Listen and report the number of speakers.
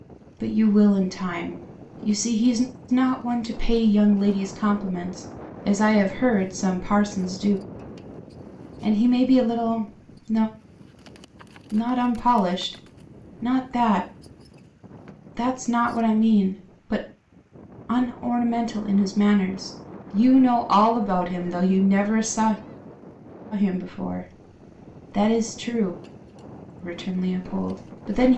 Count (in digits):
1